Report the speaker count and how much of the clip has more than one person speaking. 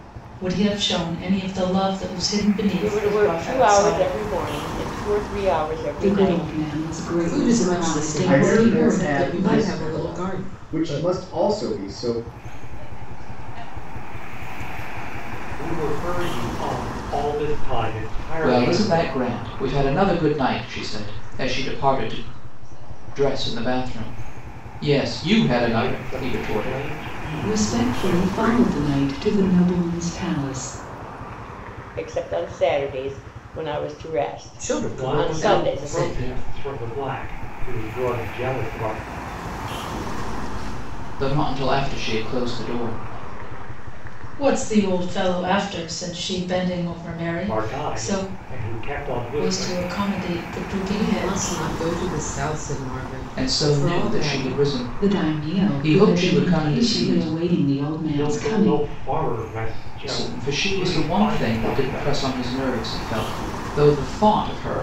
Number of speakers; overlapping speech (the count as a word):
eight, about 41%